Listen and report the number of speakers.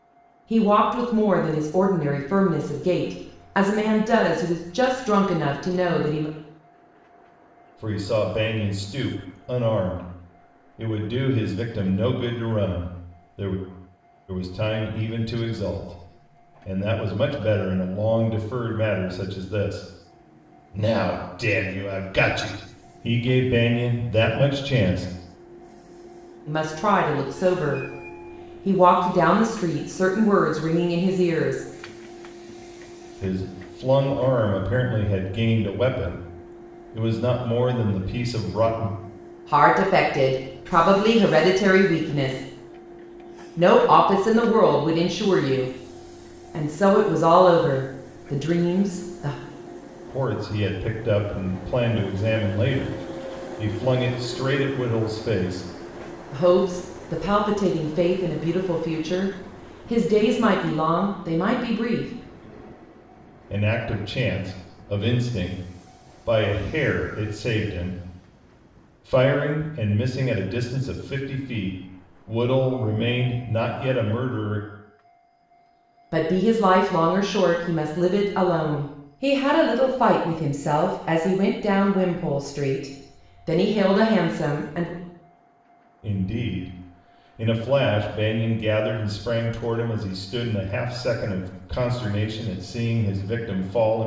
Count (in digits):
2